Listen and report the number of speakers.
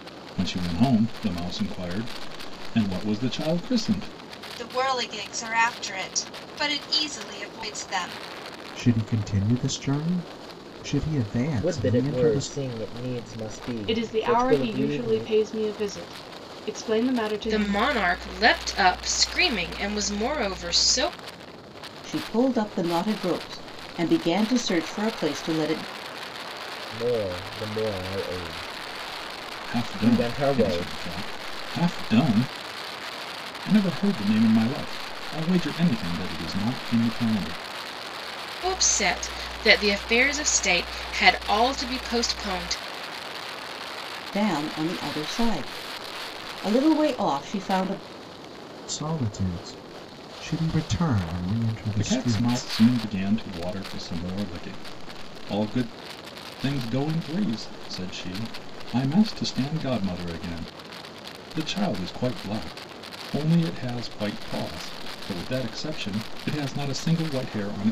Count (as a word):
seven